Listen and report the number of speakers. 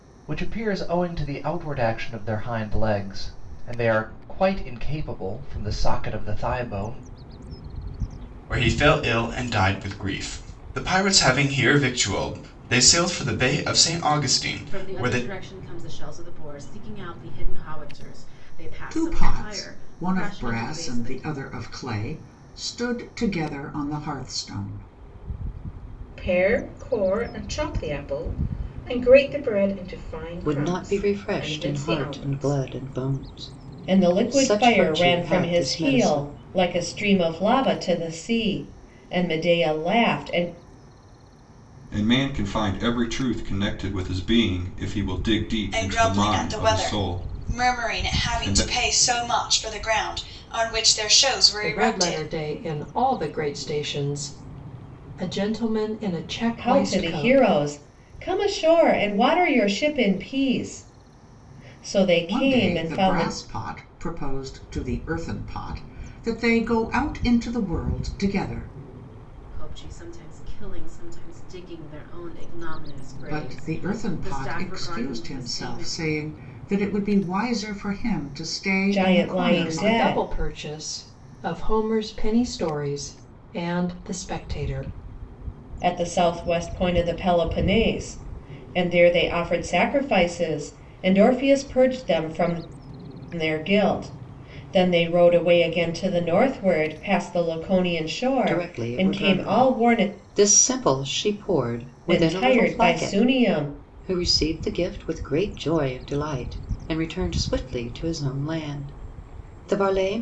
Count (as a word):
ten